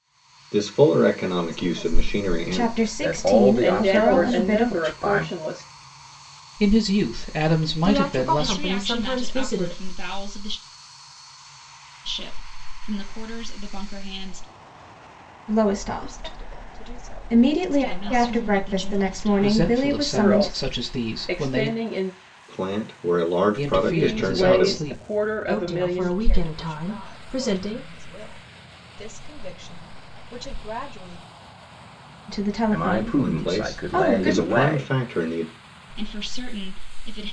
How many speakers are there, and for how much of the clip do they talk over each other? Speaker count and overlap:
8, about 48%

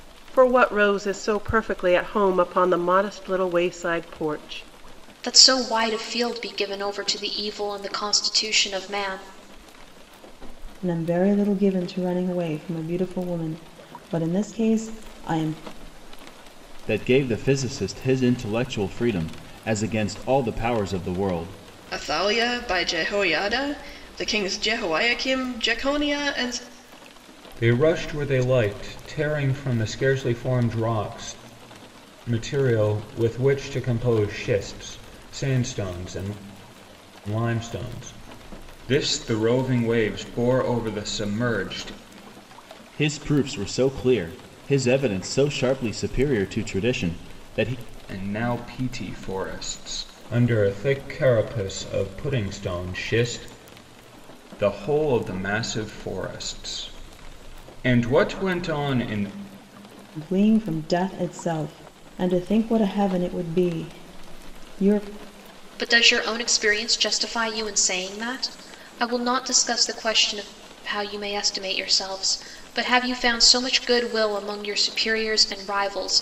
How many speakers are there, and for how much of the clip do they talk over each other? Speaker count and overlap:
6, no overlap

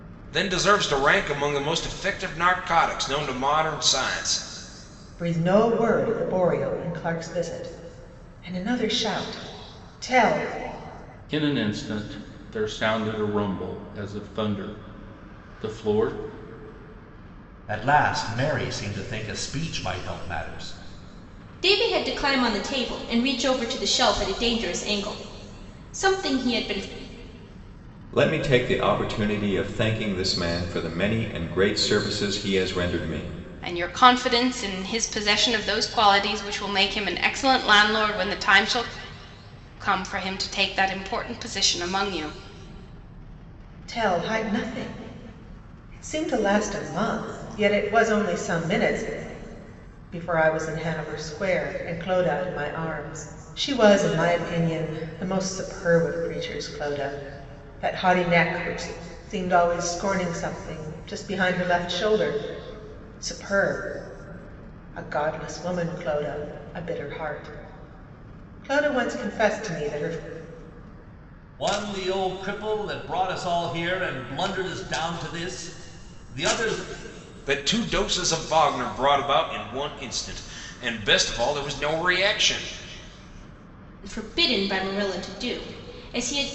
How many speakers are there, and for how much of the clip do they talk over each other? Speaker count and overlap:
7, no overlap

